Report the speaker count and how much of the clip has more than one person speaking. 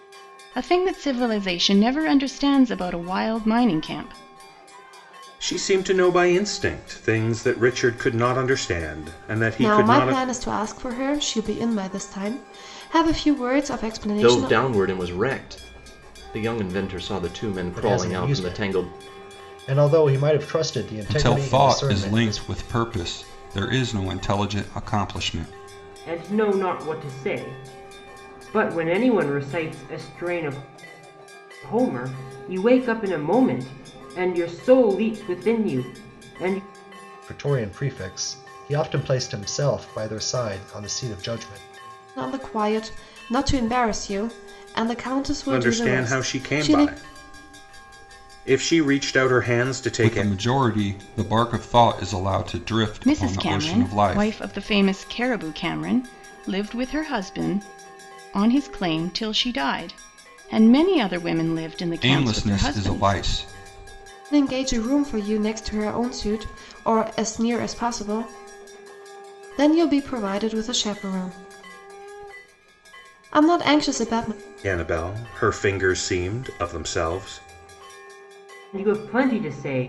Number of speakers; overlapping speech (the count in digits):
7, about 10%